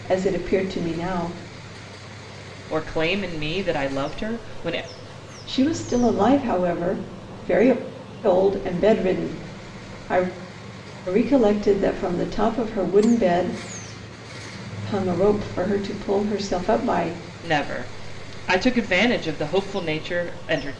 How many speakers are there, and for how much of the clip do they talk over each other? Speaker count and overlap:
two, no overlap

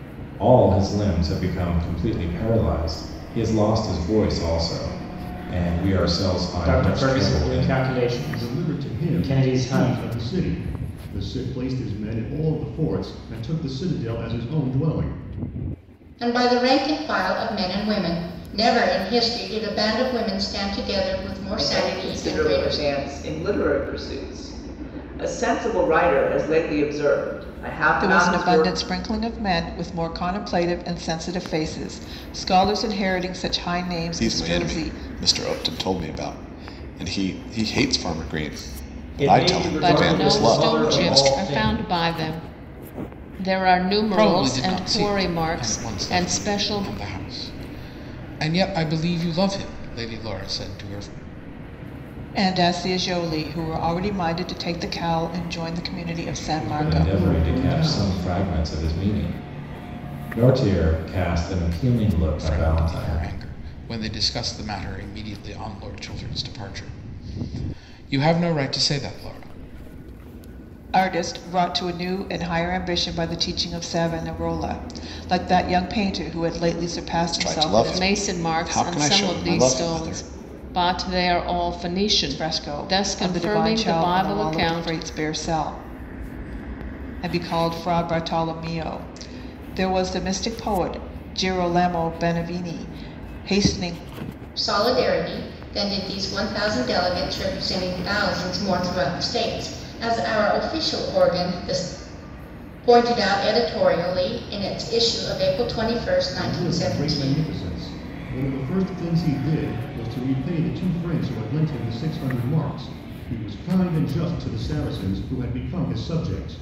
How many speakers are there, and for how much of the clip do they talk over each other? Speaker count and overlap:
ten, about 18%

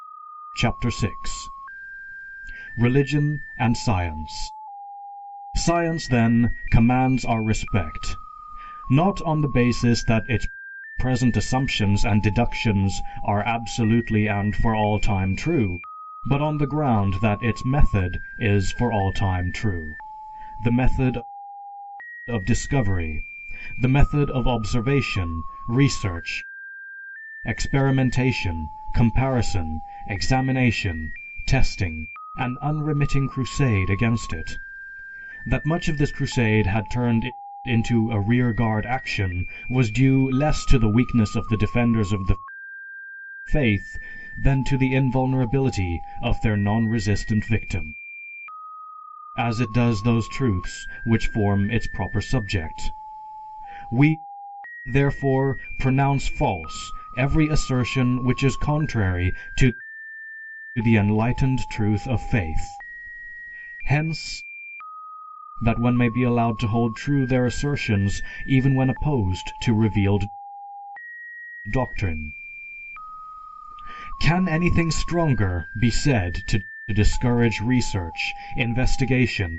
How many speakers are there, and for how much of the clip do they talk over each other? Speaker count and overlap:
one, no overlap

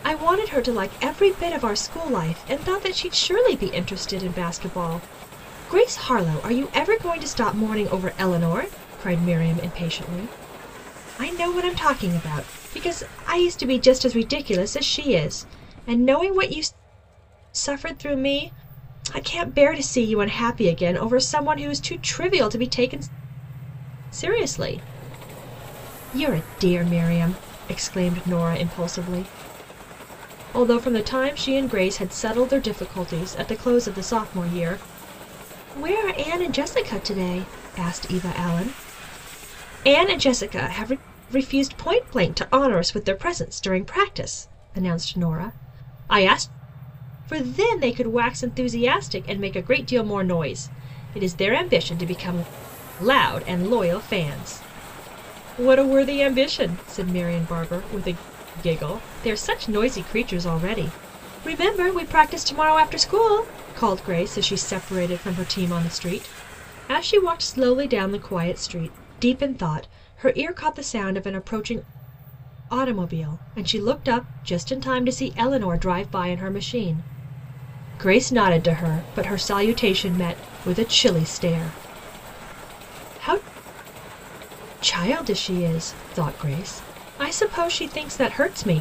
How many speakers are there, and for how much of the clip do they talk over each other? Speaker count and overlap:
one, no overlap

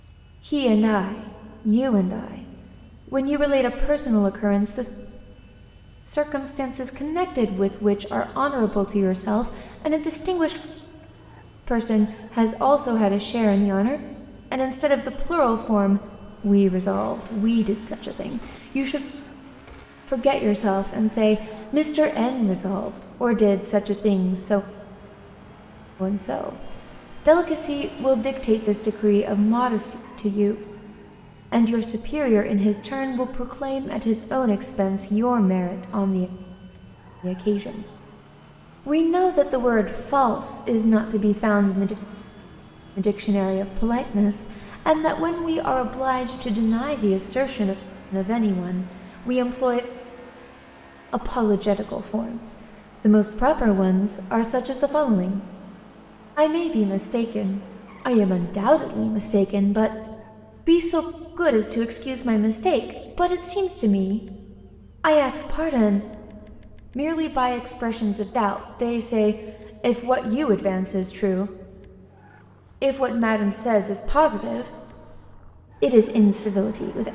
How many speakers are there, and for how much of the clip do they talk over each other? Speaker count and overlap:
one, no overlap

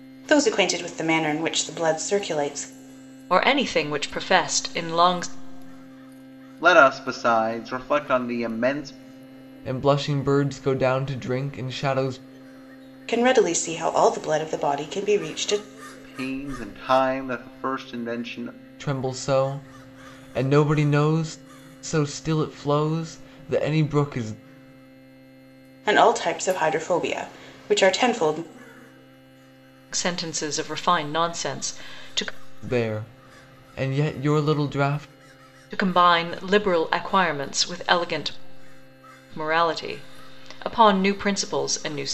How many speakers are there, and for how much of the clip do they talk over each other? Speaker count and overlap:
four, no overlap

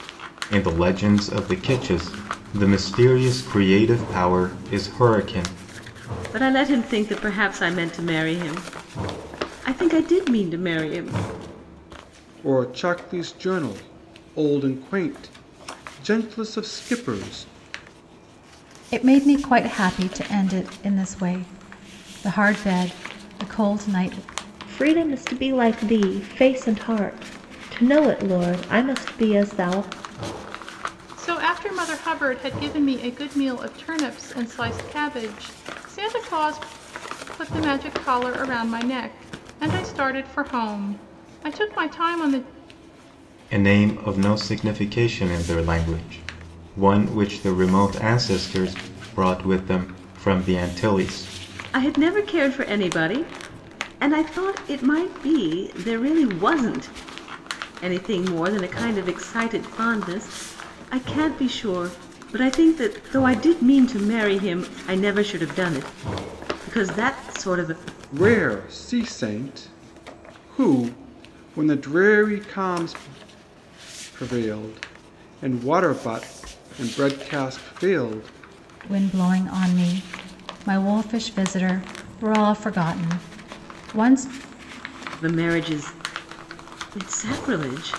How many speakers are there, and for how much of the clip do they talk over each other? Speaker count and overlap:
six, no overlap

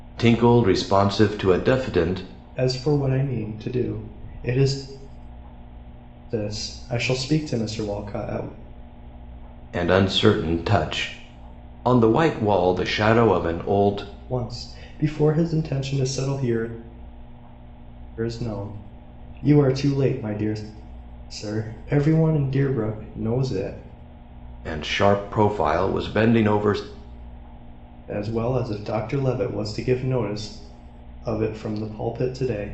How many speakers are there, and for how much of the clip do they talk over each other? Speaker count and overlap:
two, no overlap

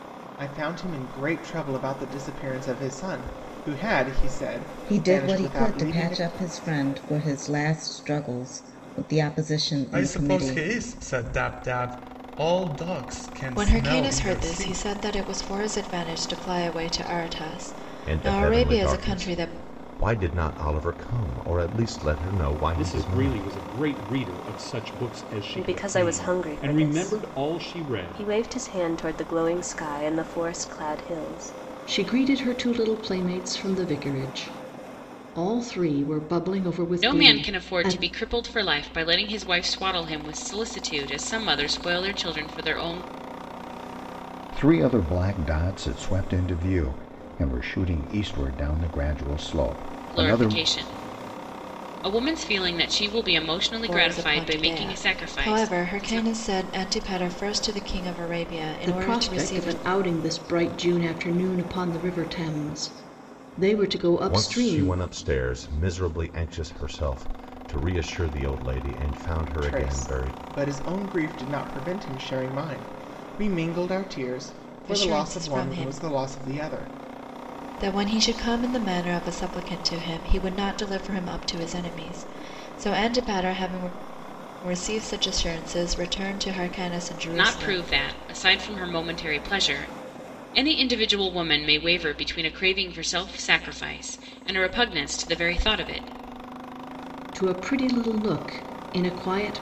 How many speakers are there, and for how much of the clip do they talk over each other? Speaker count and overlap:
ten, about 17%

